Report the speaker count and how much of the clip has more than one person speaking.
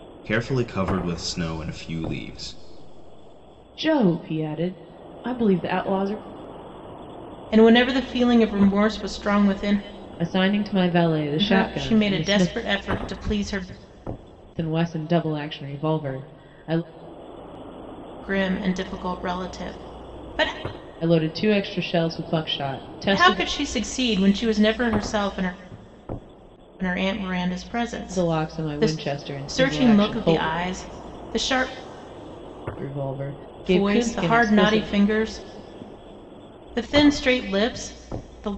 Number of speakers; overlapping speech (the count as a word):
three, about 12%